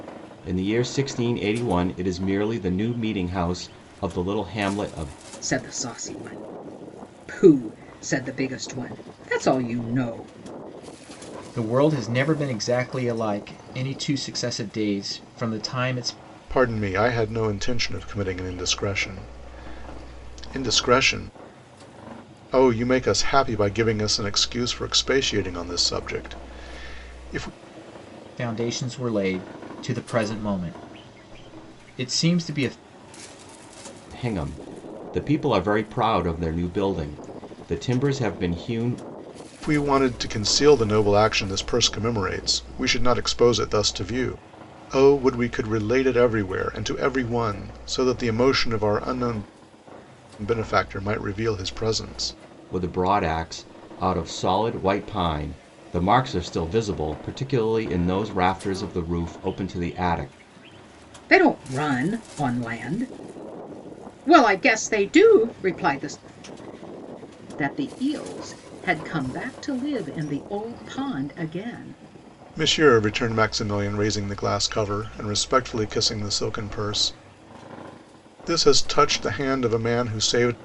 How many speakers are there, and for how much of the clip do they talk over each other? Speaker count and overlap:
four, no overlap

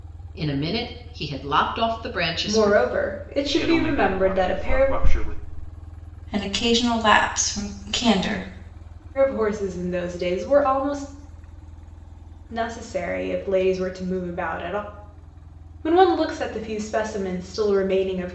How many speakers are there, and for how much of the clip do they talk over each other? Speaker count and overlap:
four, about 10%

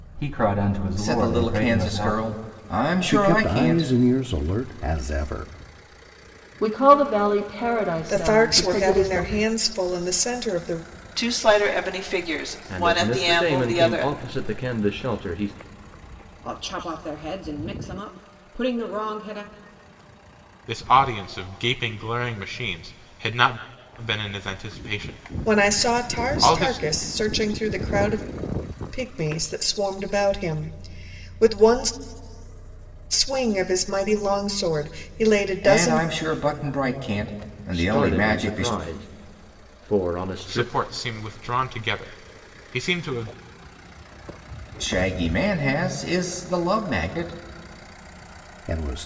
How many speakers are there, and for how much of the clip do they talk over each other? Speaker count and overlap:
nine, about 16%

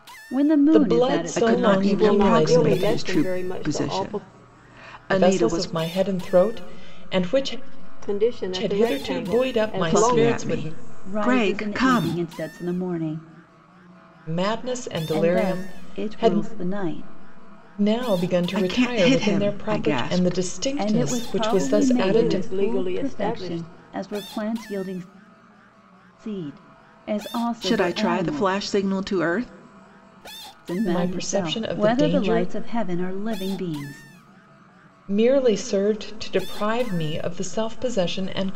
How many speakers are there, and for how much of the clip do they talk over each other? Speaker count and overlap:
four, about 42%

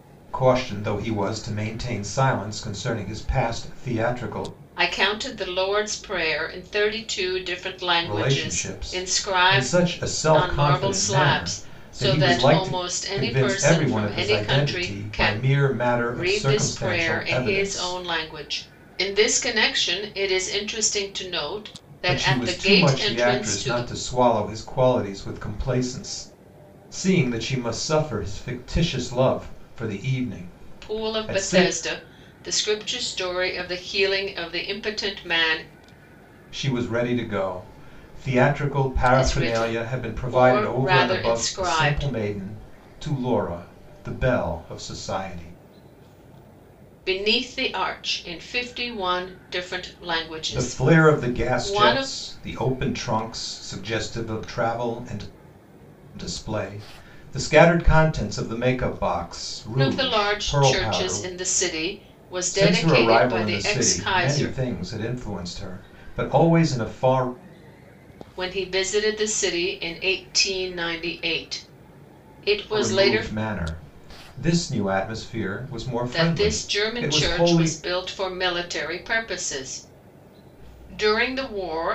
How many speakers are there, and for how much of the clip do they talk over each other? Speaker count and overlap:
two, about 27%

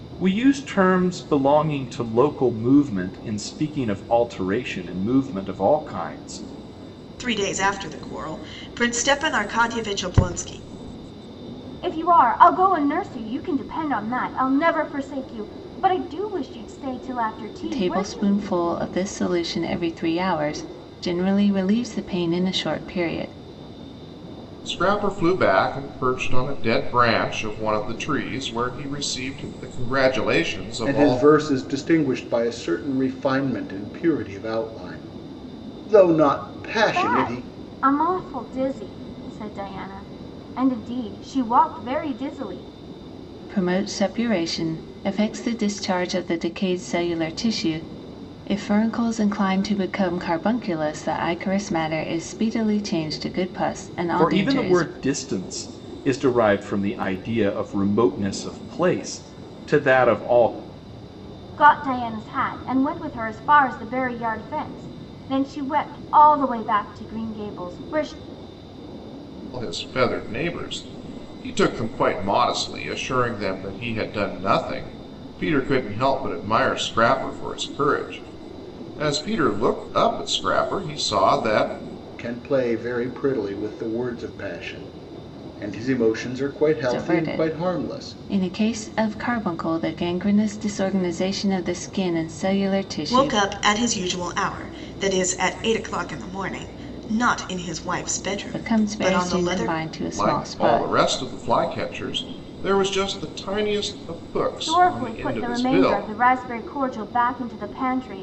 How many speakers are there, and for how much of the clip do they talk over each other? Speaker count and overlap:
six, about 8%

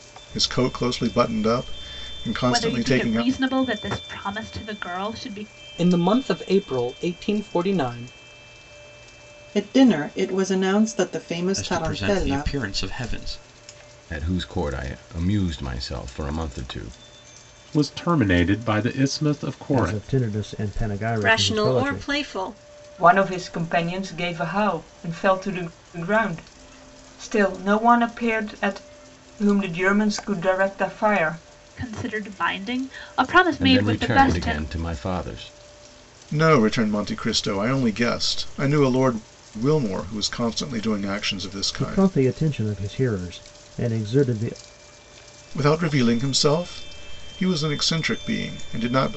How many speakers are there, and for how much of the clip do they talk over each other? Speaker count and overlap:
ten, about 10%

